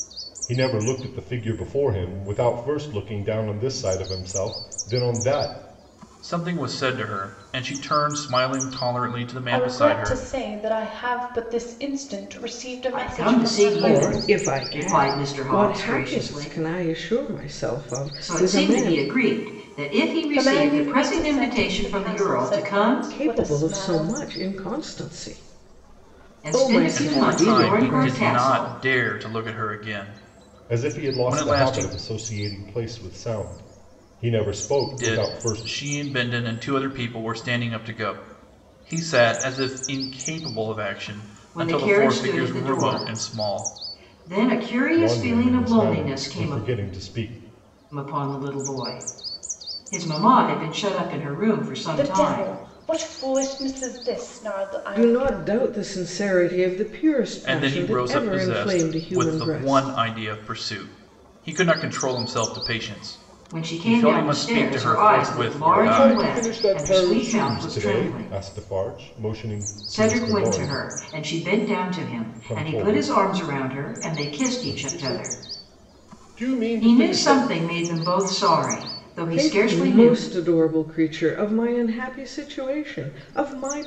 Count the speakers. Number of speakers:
5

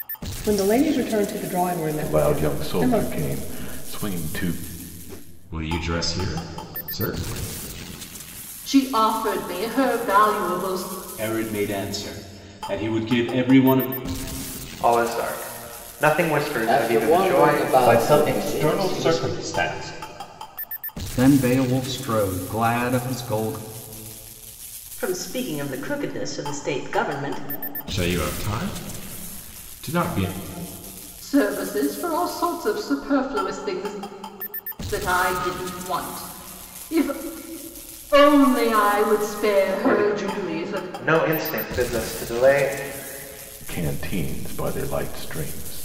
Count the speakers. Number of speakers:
10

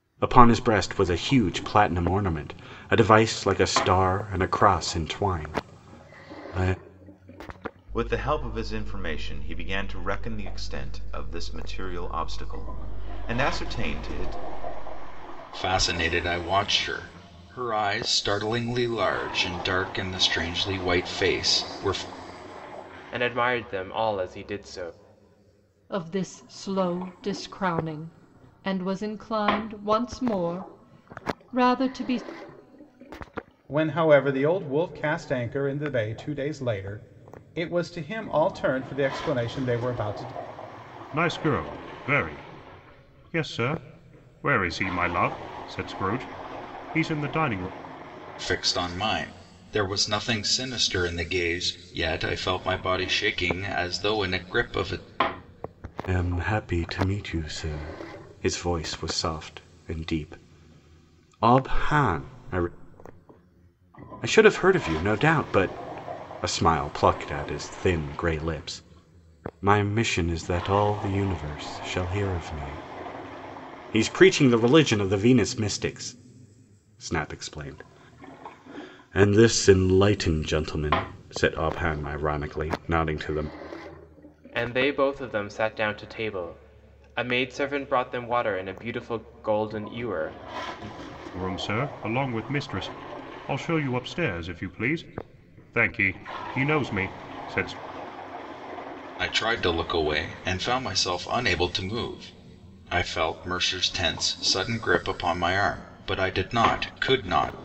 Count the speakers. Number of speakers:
7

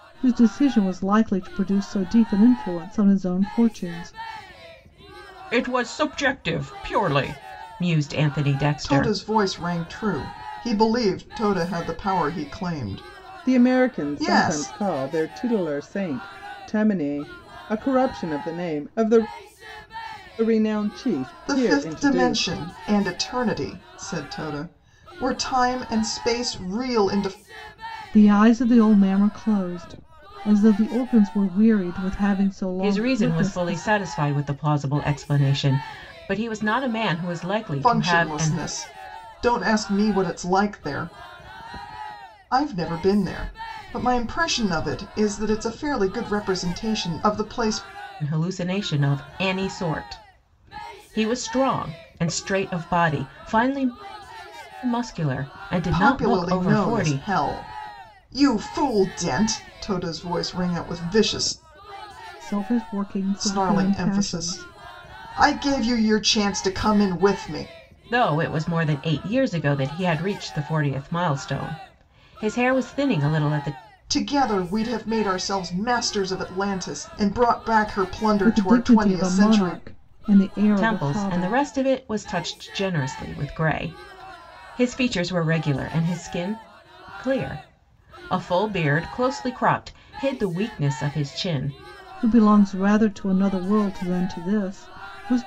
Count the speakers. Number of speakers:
3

